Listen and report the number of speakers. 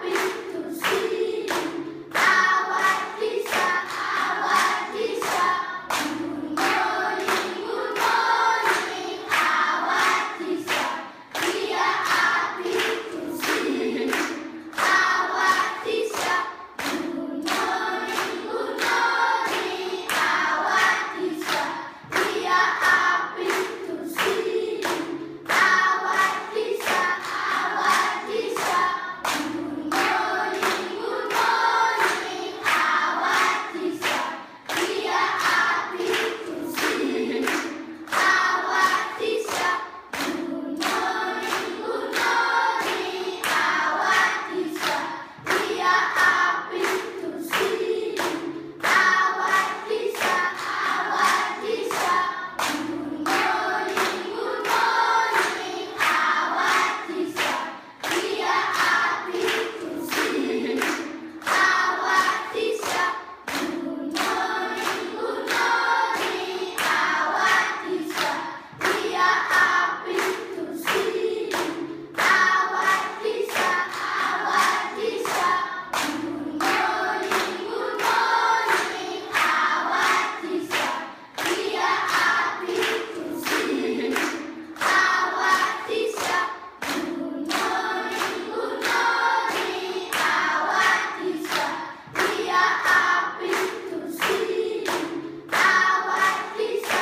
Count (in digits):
0